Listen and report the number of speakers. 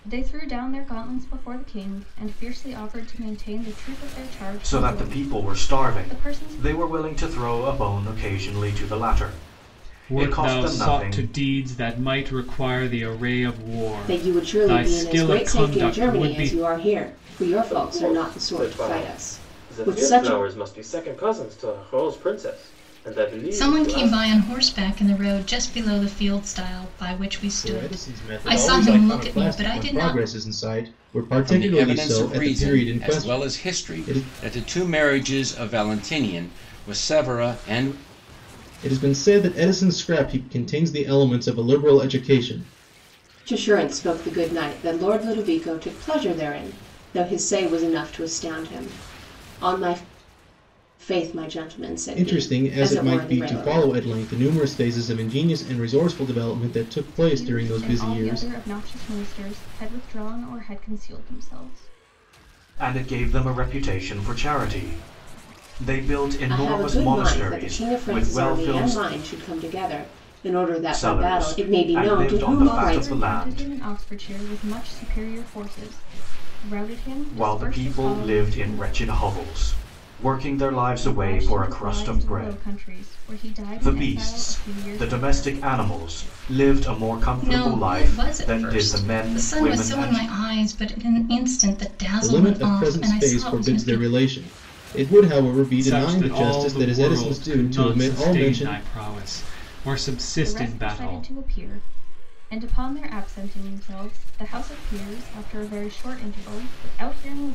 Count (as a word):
eight